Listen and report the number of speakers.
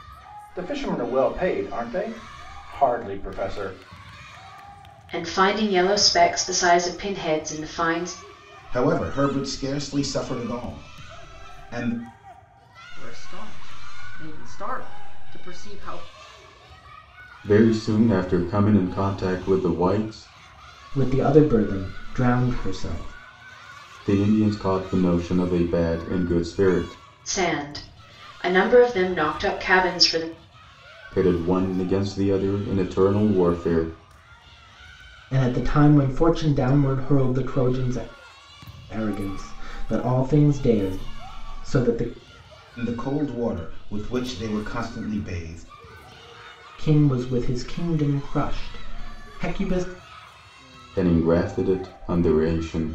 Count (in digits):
6